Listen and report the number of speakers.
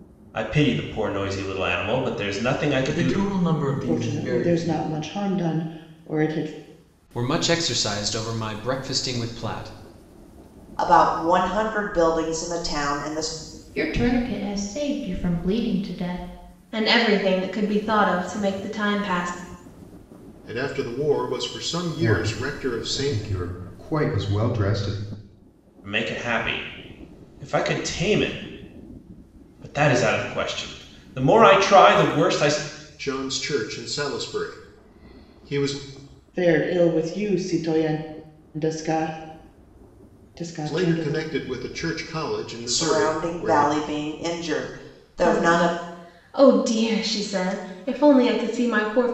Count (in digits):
9